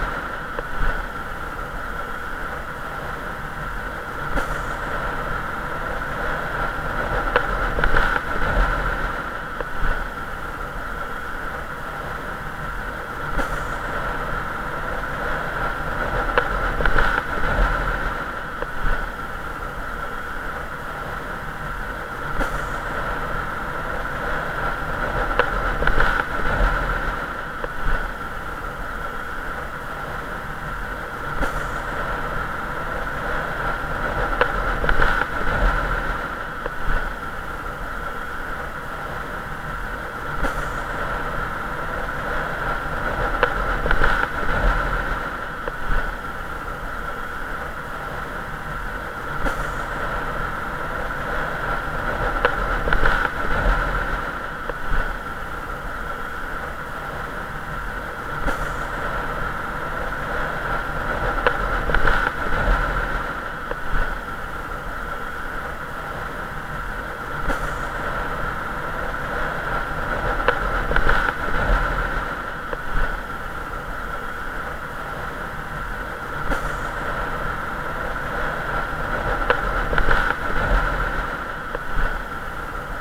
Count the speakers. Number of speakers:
0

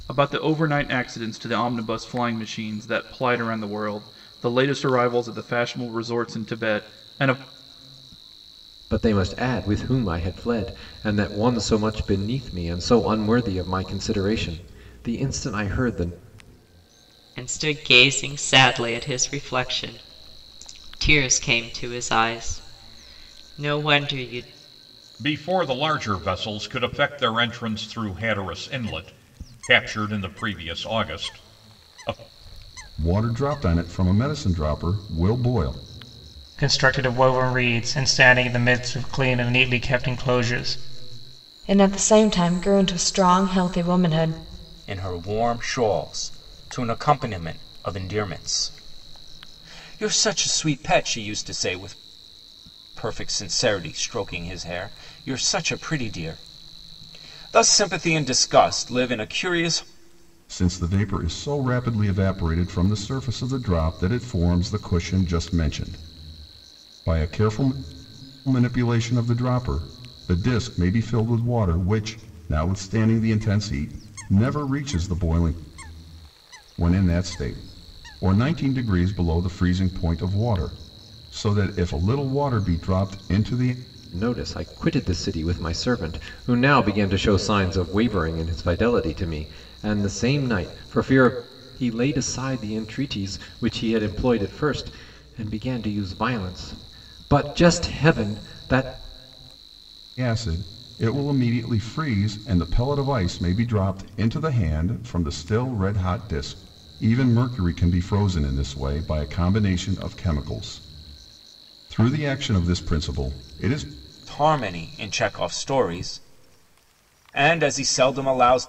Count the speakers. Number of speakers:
8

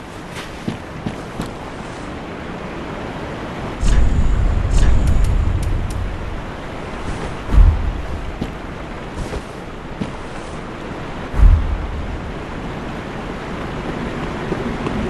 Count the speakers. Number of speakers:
0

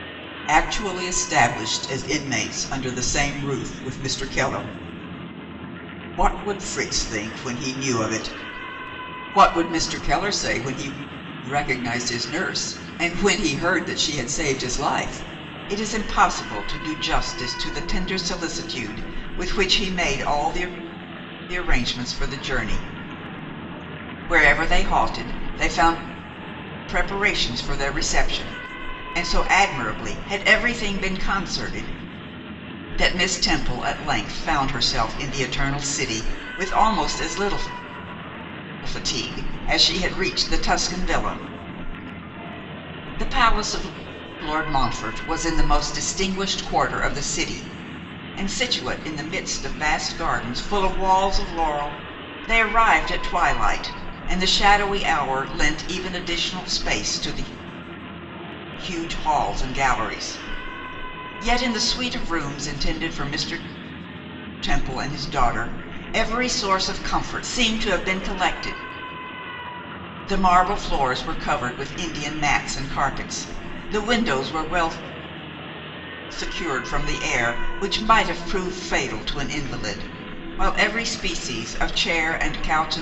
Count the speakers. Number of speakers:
1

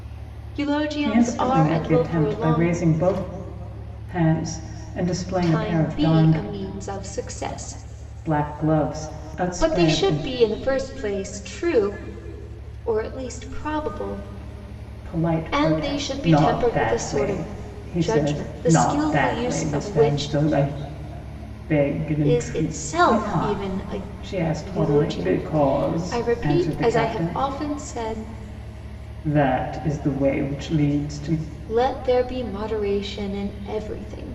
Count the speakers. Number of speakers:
2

